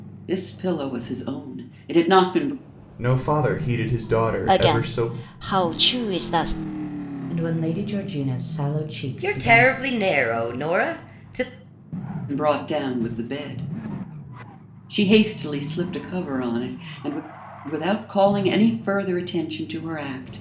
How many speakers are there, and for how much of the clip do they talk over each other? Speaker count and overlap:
5, about 6%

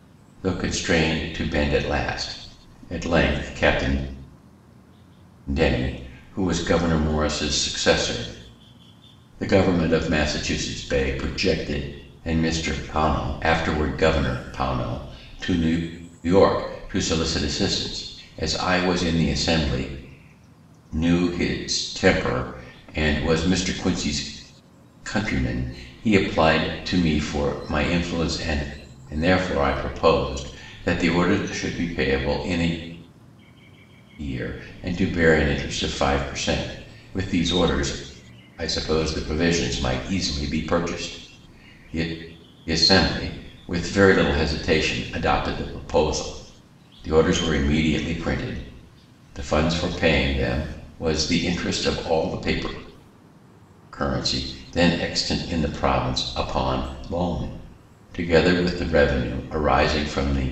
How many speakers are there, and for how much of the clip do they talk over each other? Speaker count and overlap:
1, no overlap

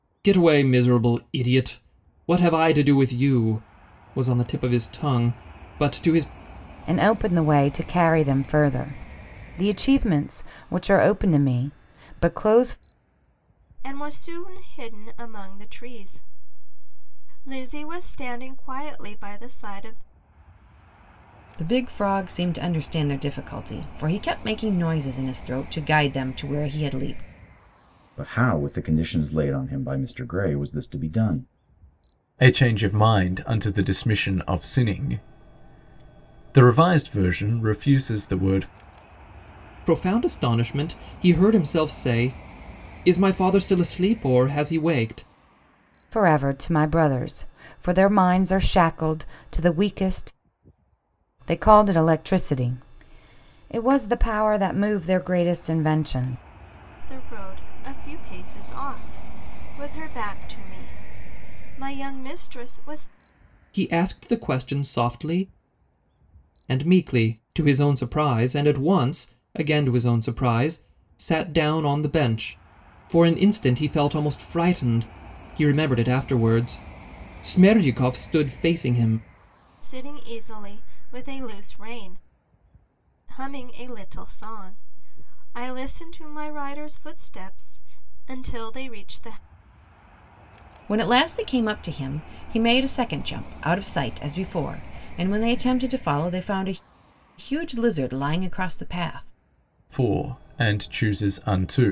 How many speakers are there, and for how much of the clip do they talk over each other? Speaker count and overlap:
6, no overlap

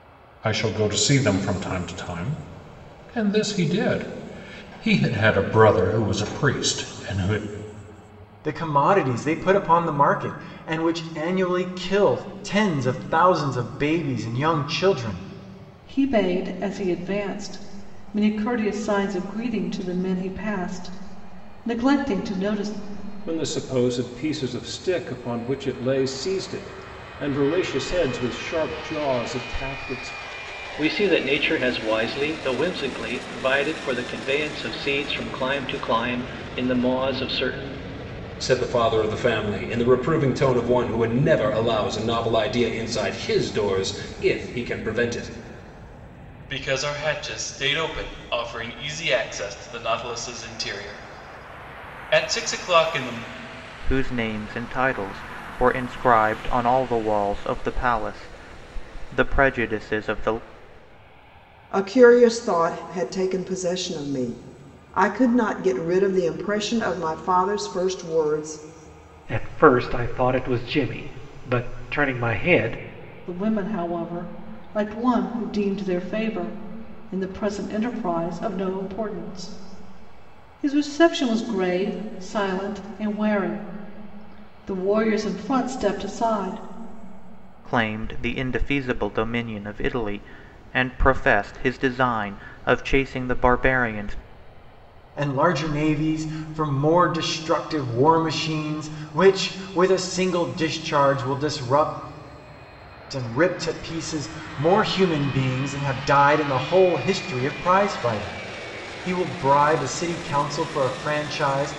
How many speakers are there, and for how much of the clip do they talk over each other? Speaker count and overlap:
10, no overlap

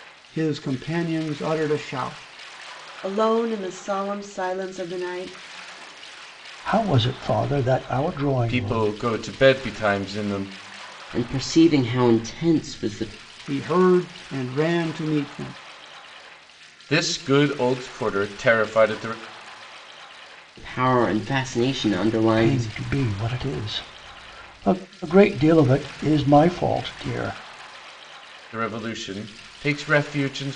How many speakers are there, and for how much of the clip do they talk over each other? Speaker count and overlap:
5, about 3%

